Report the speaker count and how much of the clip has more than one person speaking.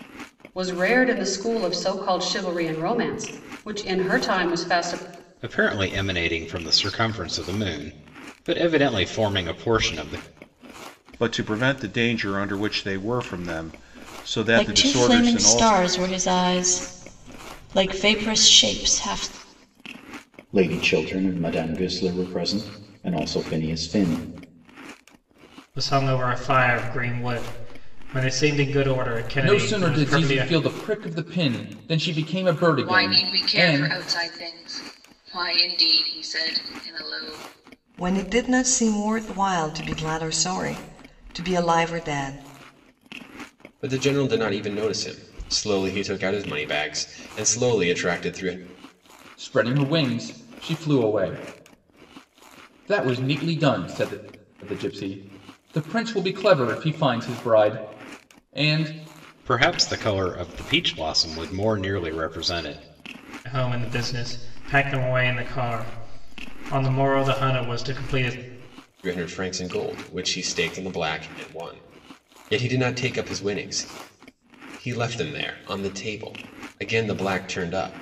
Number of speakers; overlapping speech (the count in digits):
10, about 5%